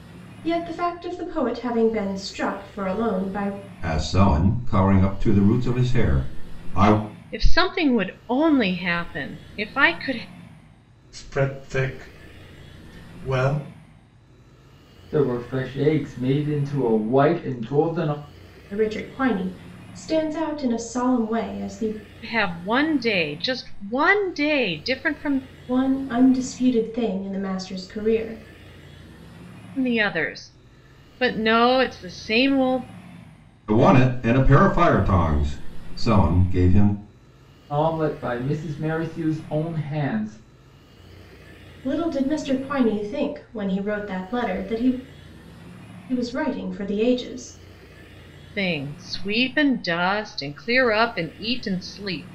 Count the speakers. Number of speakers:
five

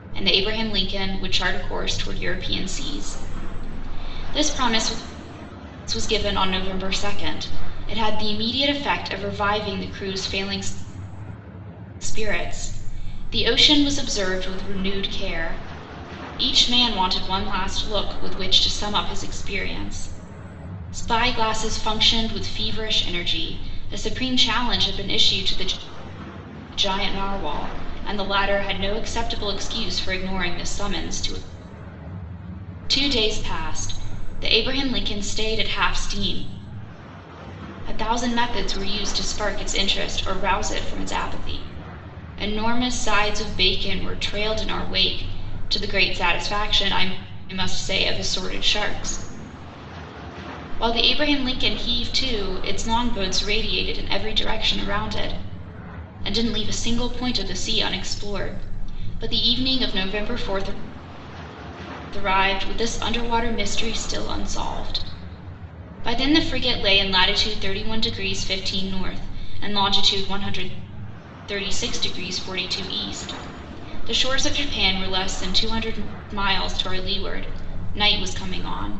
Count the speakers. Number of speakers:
one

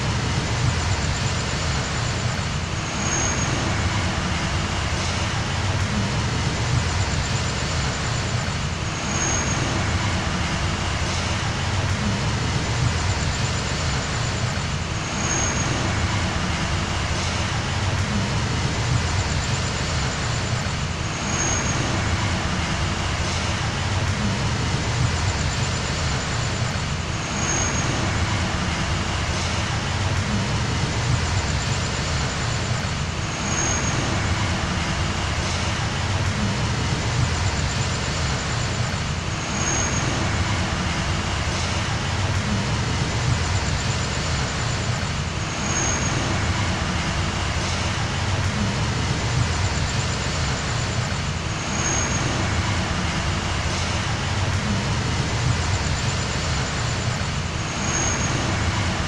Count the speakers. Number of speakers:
zero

